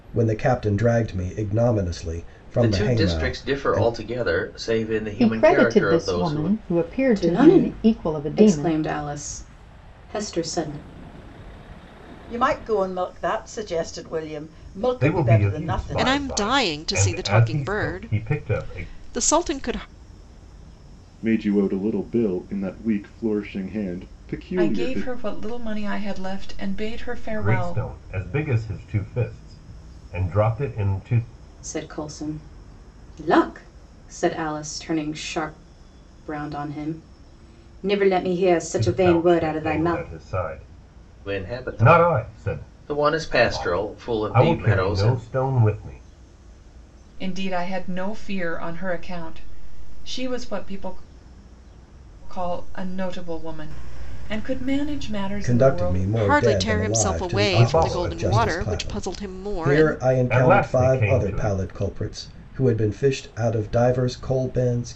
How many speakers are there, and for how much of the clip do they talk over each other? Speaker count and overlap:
9, about 31%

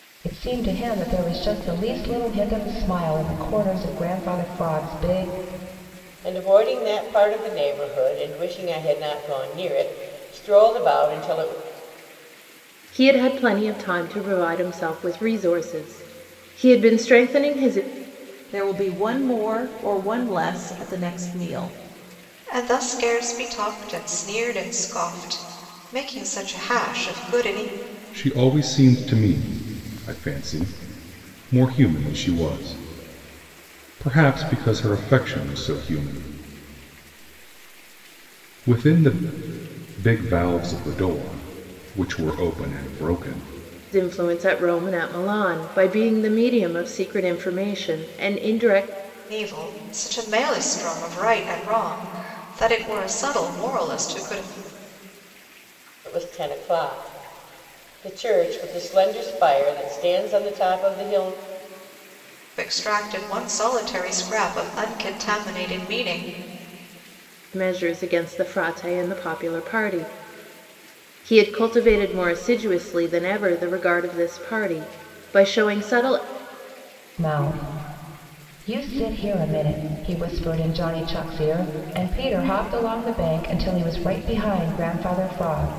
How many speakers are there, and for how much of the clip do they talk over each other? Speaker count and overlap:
6, no overlap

